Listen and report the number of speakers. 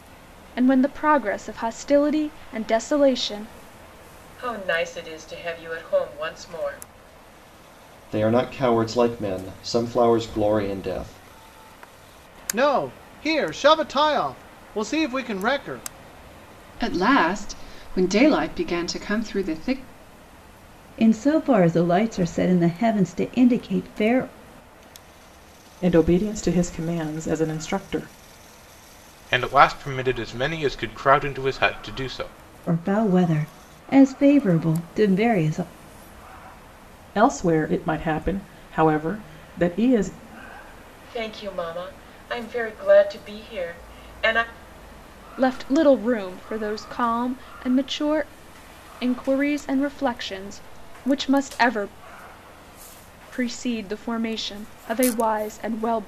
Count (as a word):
eight